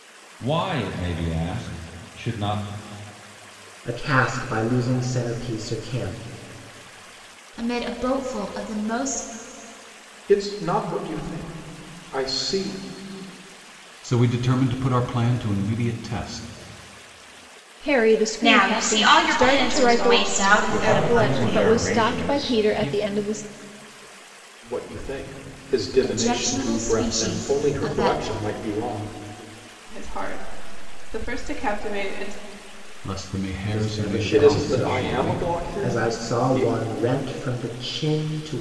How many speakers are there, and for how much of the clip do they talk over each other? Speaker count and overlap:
ten, about 25%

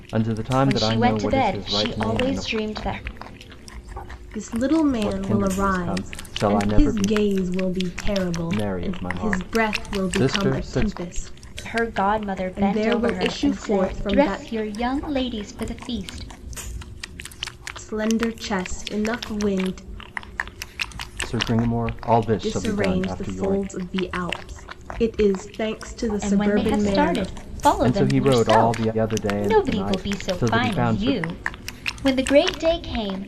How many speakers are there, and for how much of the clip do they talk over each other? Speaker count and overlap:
three, about 45%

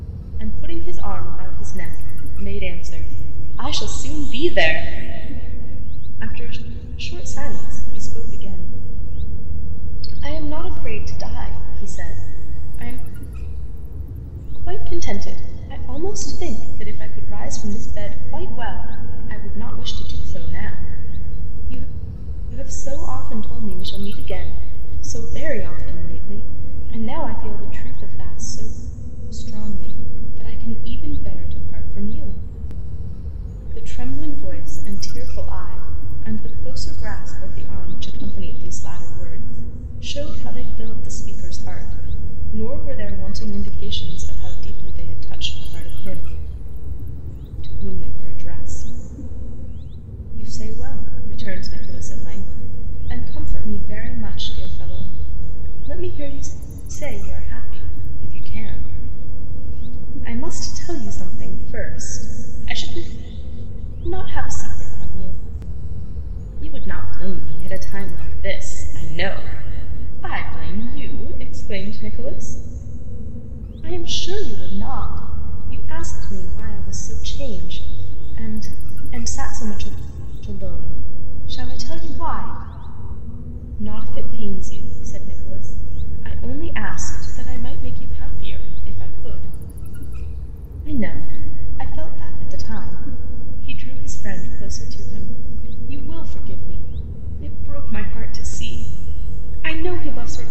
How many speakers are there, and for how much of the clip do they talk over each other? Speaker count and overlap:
one, no overlap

